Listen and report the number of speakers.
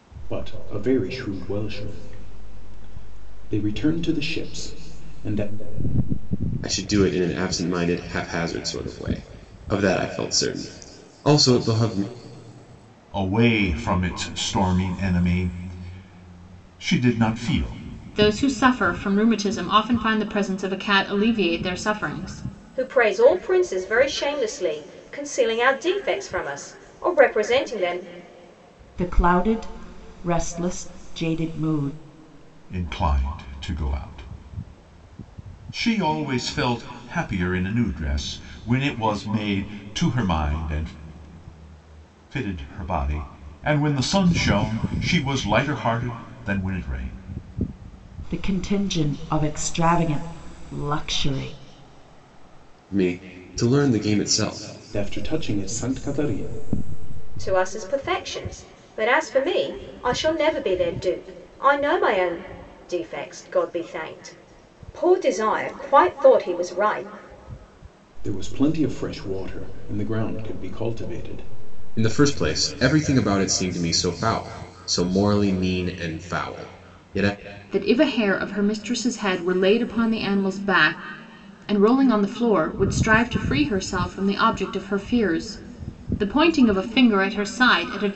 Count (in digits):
6